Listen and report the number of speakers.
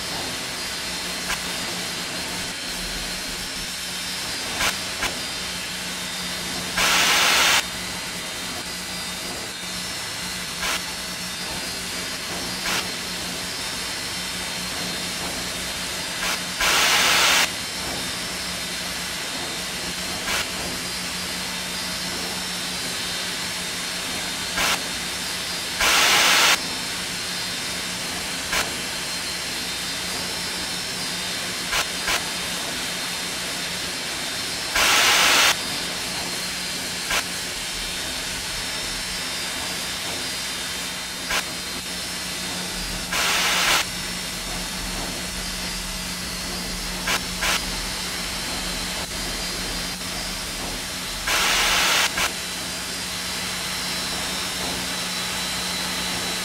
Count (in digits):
0